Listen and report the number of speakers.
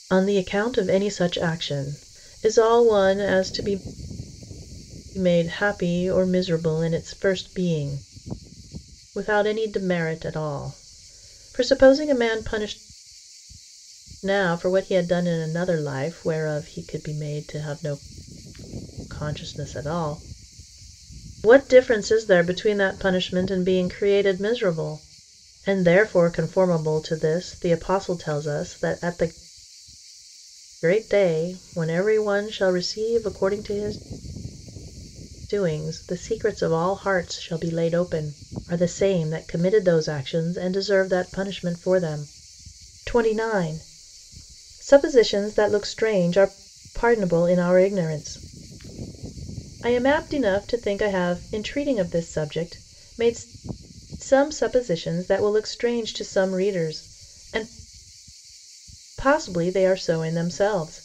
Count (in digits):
1